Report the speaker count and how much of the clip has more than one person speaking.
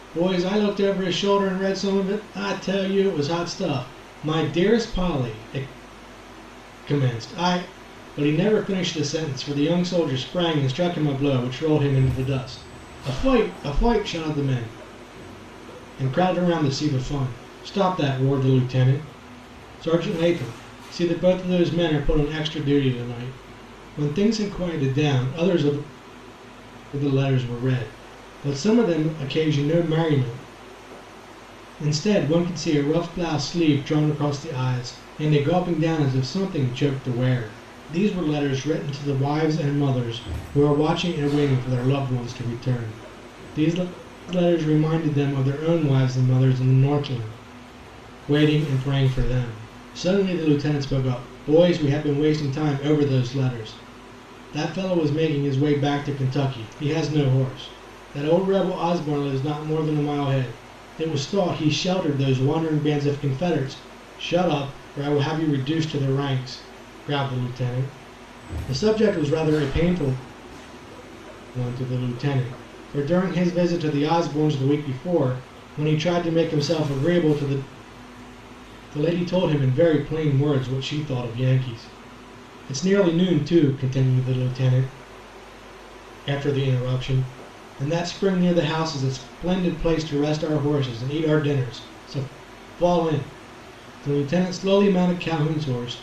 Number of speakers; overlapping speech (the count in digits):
1, no overlap